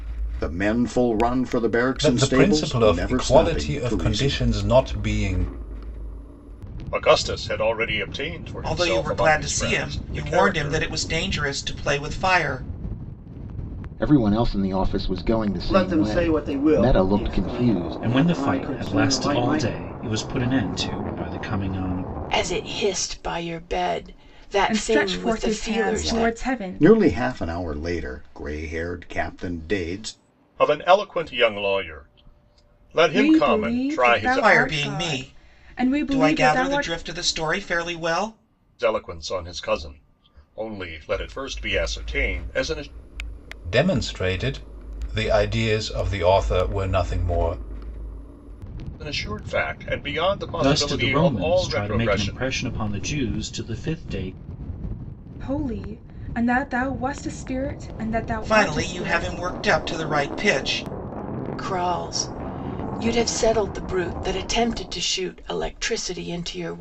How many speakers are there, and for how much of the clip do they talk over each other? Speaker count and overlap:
9, about 27%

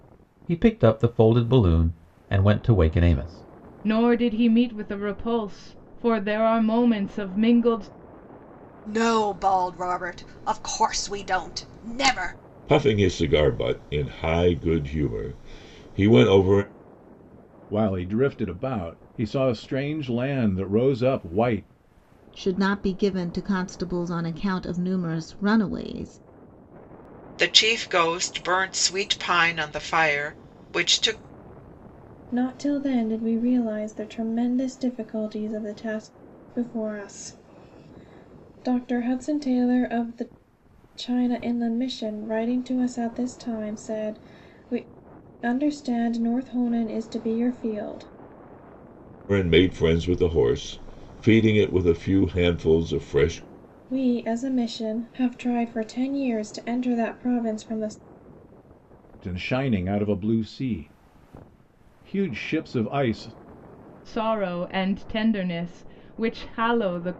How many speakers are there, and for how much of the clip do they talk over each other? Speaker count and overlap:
8, no overlap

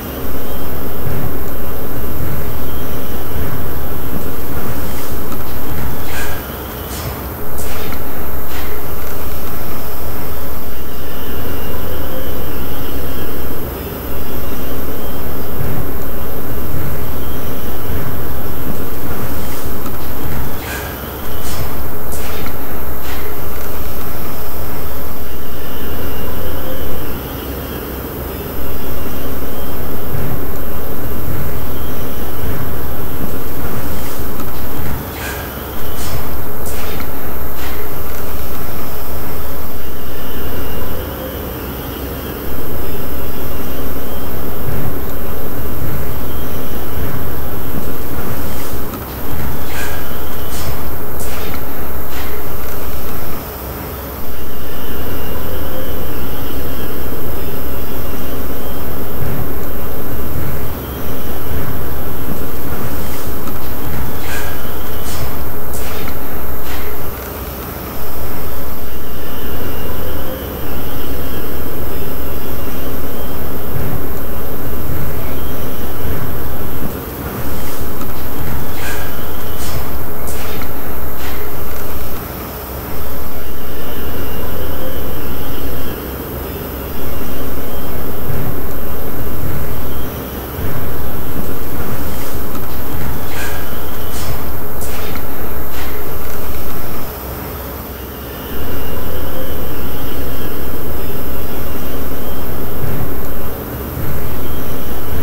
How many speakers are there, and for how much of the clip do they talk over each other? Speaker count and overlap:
1, no overlap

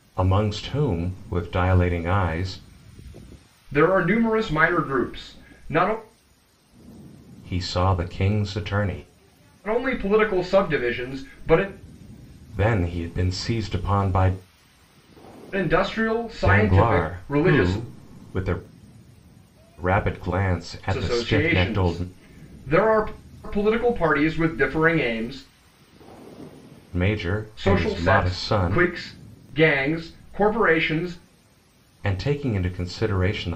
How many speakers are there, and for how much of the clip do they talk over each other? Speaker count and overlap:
2, about 11%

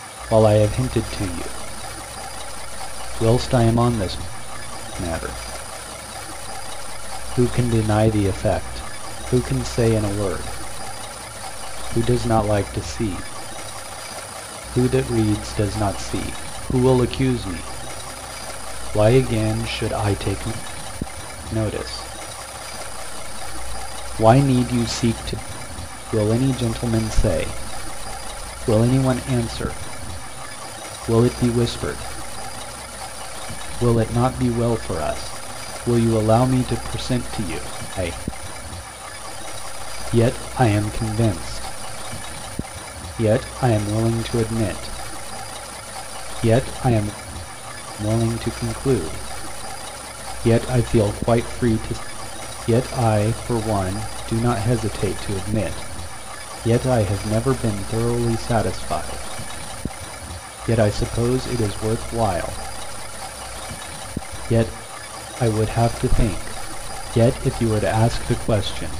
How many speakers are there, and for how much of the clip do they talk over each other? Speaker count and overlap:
1, no overlap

